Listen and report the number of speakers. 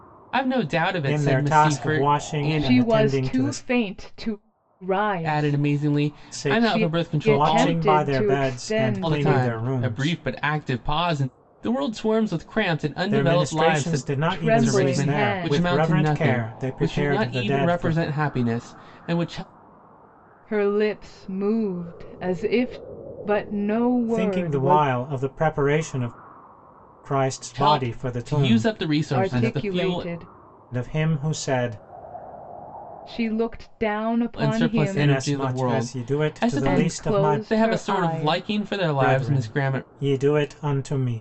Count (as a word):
three